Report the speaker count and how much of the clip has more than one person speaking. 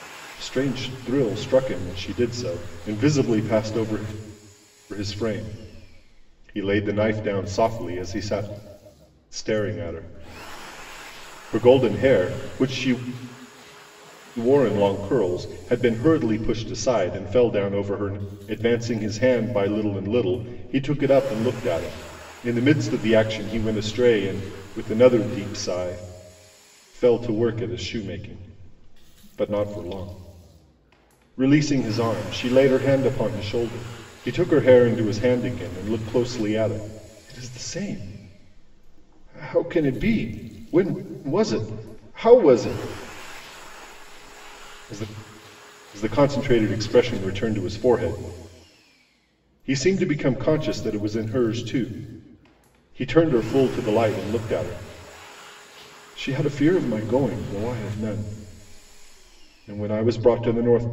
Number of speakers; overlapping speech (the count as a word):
one, no overlap